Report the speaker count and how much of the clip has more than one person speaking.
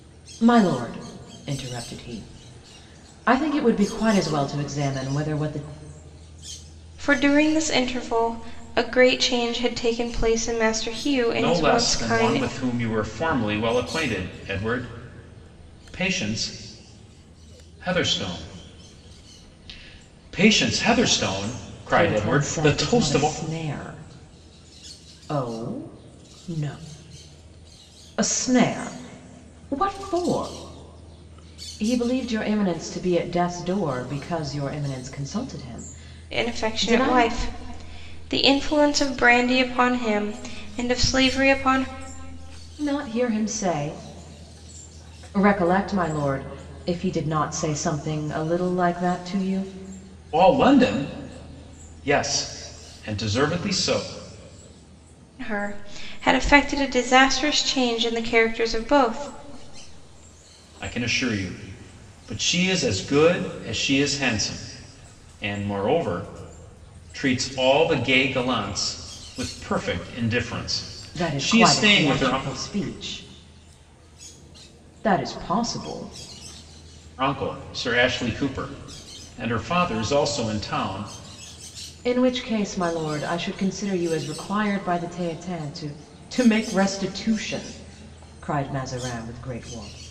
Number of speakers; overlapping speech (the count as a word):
three, about 5%